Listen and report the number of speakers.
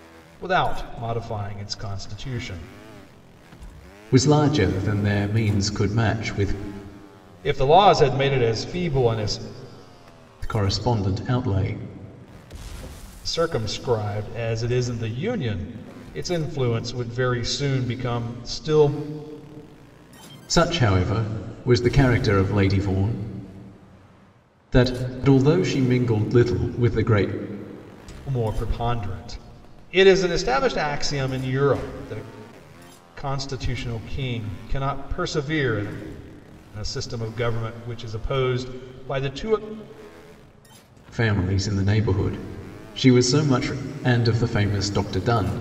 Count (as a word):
two